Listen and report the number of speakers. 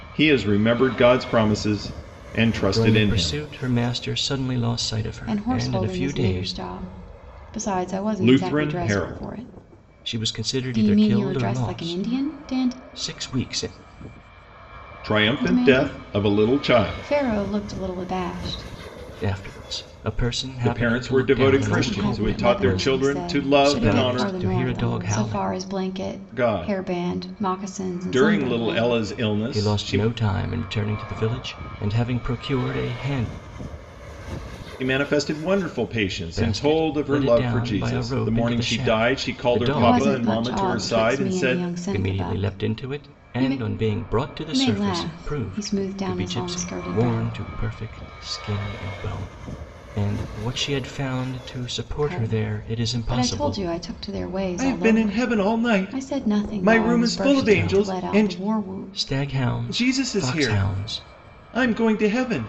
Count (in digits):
3